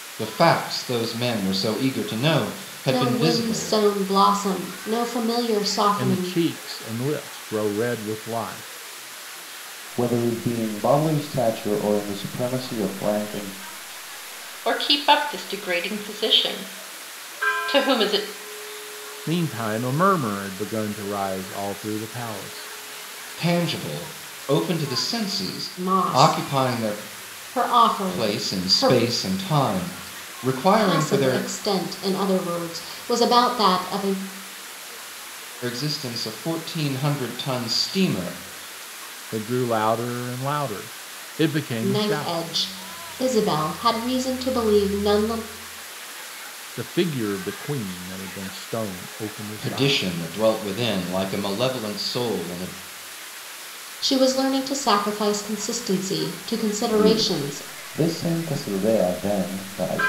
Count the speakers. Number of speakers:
five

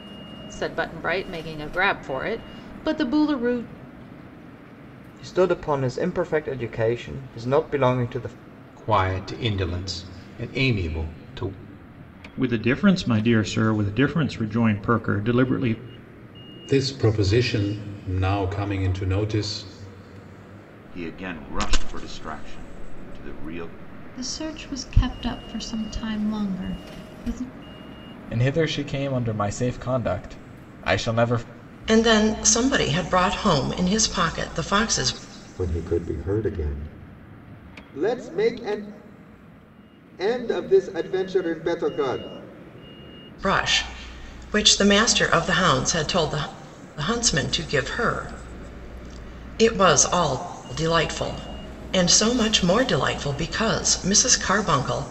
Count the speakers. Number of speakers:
ten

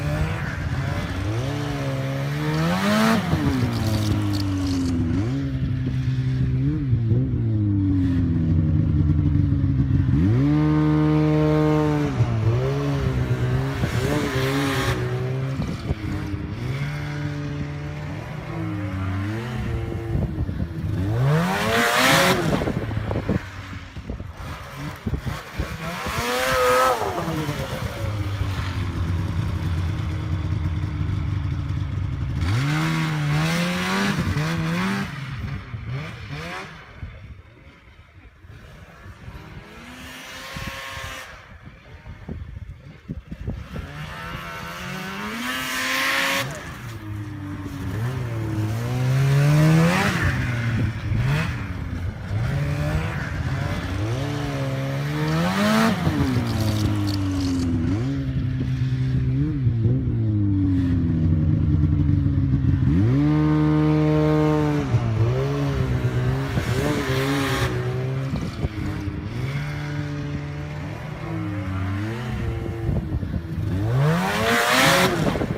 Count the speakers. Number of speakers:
zero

